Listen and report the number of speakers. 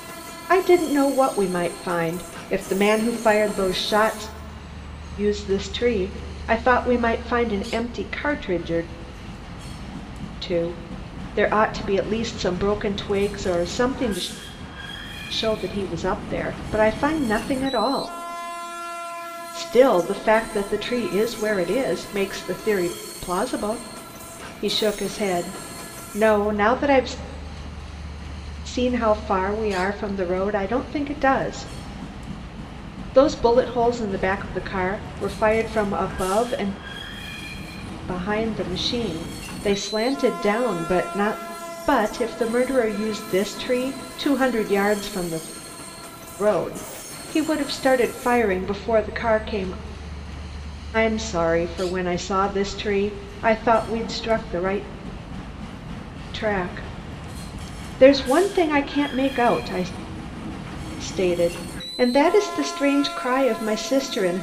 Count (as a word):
one